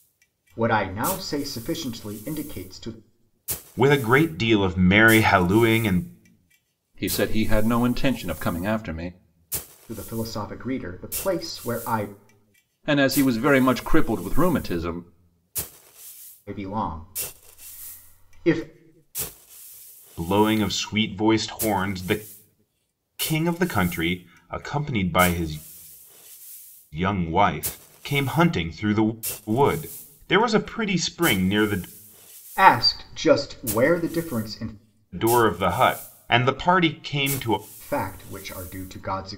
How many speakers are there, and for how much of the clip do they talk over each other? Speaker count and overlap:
three, no overlap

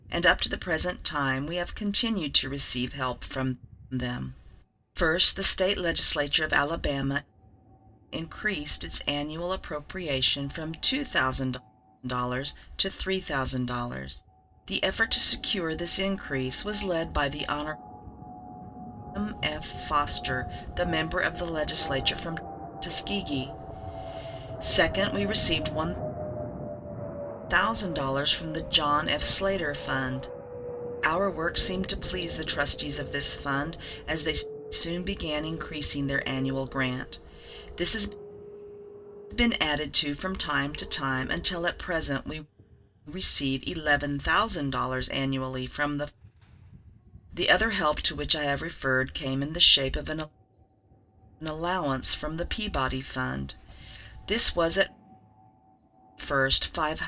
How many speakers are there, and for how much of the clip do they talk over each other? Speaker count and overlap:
one, no overlap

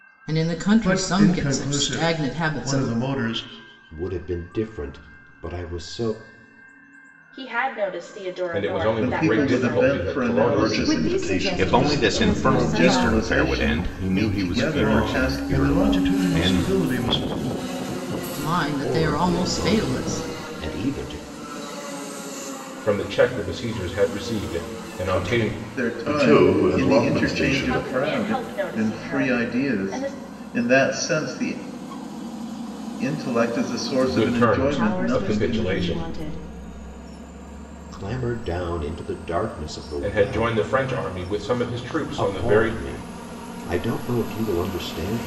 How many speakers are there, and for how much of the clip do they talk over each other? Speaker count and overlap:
nine, about 44%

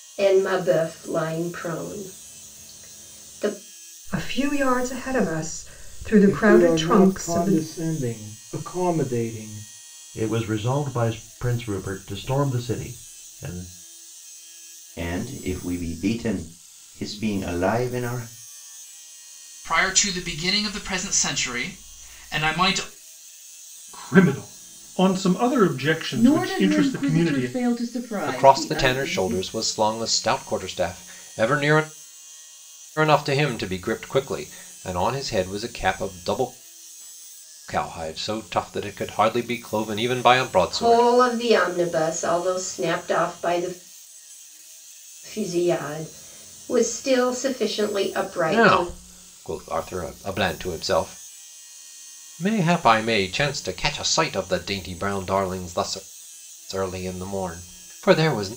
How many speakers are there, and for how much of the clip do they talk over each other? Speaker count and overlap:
nine, about 8%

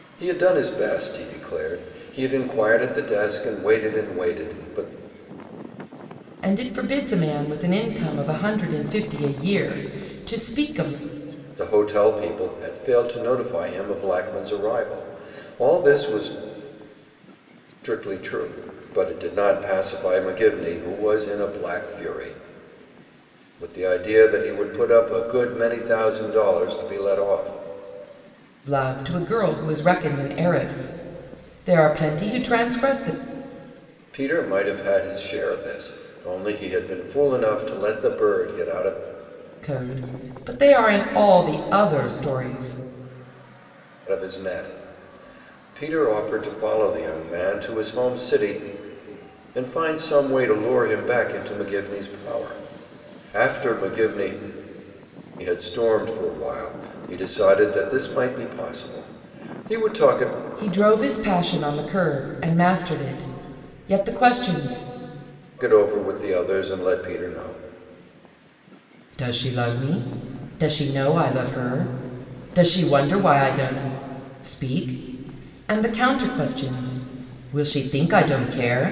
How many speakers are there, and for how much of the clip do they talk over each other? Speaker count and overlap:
two, no overlap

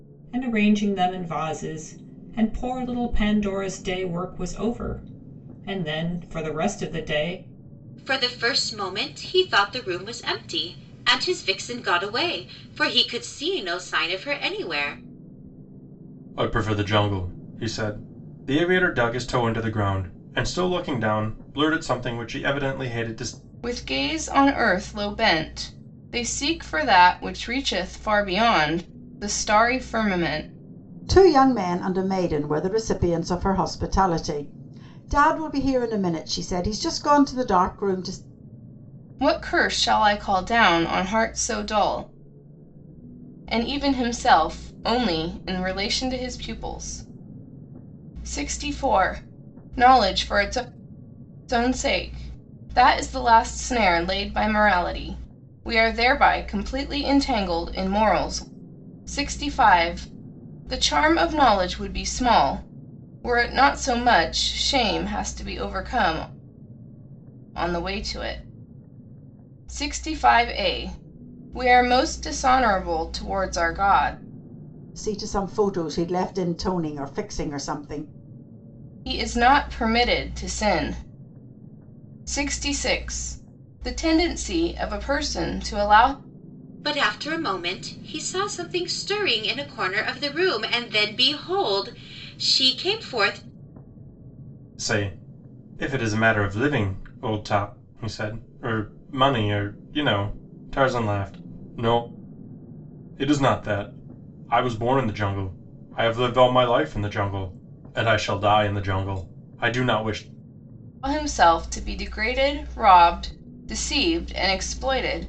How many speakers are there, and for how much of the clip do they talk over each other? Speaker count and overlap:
five, no overlap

